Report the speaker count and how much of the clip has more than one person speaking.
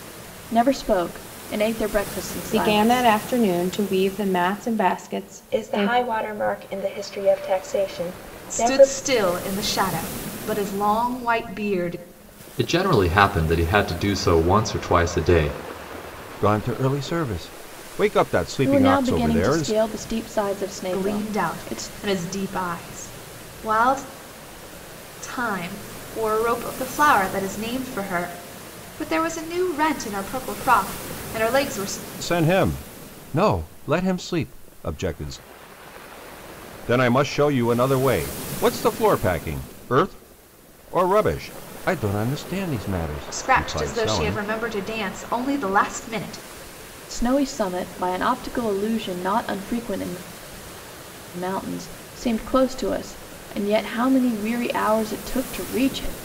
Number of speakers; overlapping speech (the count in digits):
6, about 9%